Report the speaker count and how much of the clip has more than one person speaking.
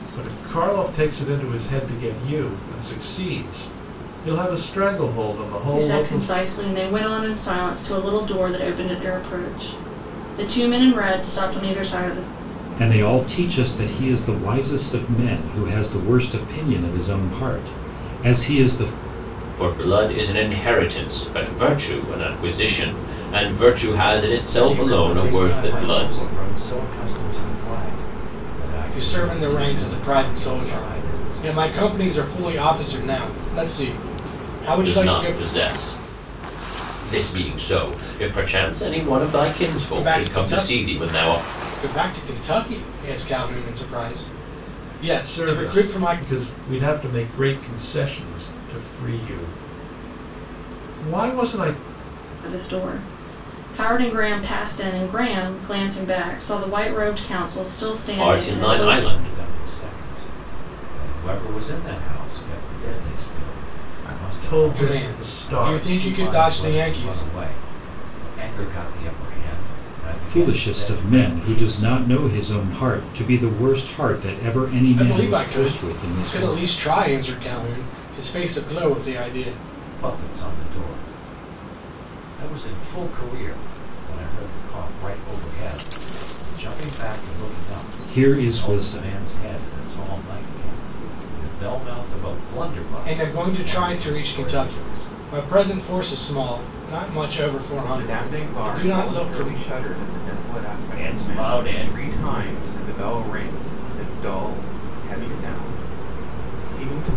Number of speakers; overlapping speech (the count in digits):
7, about 21%